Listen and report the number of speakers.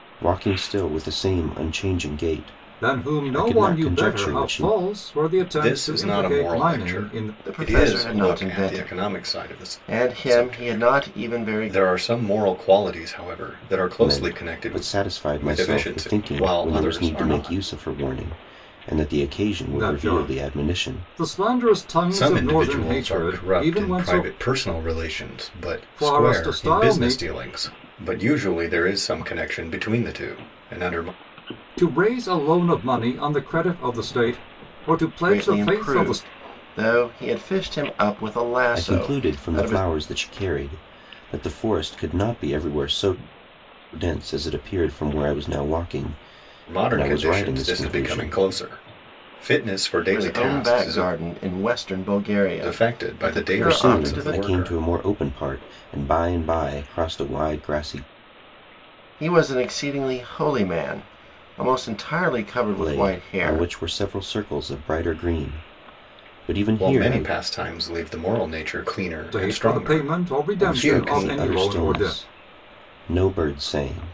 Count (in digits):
4